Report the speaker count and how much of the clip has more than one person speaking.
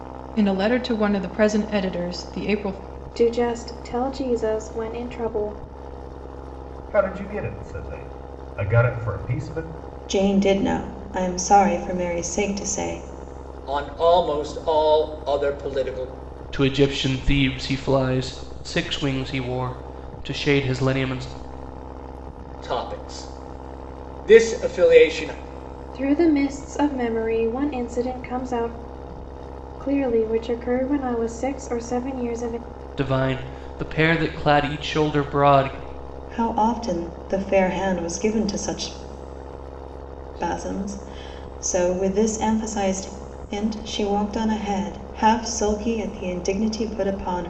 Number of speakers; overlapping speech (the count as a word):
six, no overlap